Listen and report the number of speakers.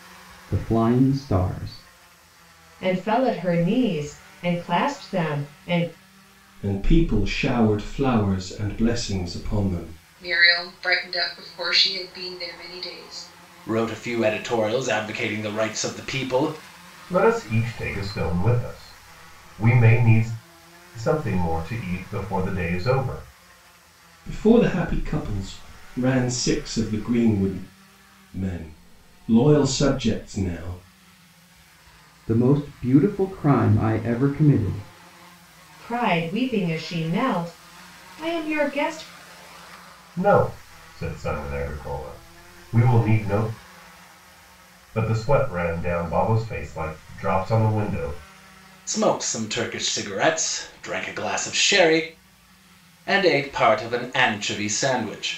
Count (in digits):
6